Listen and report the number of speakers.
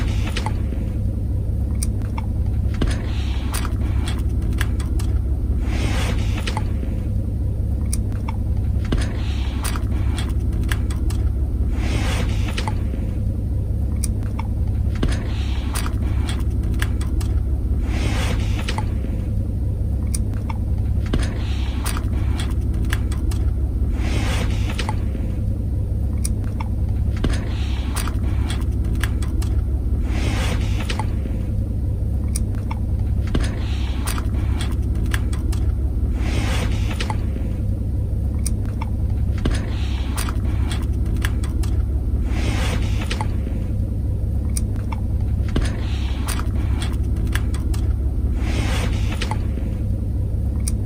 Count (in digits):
0